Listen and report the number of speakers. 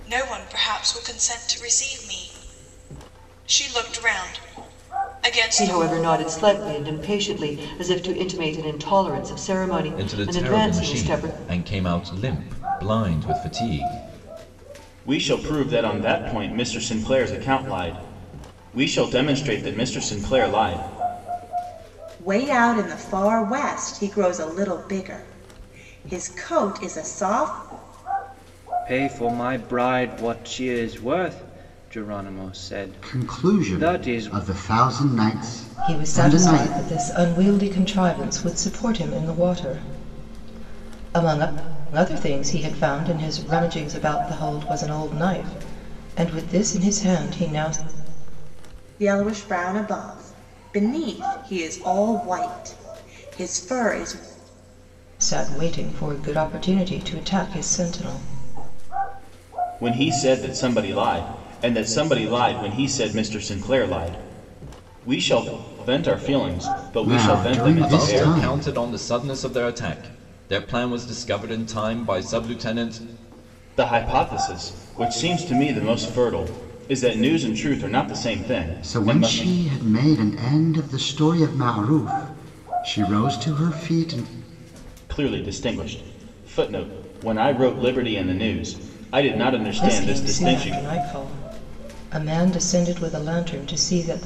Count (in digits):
8